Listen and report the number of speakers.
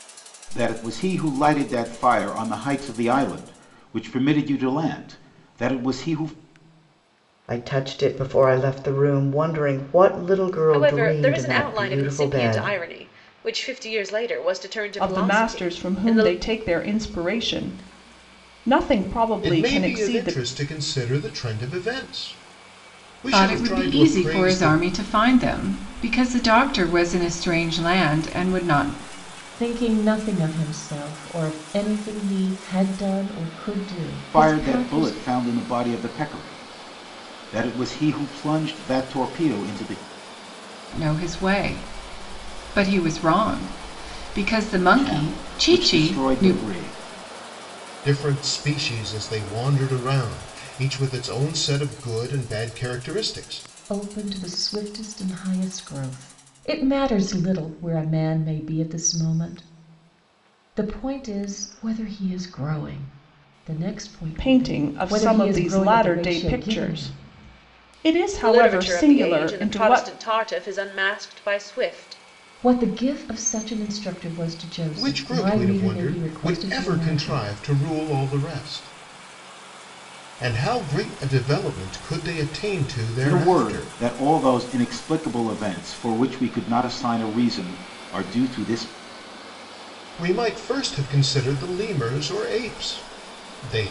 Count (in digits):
7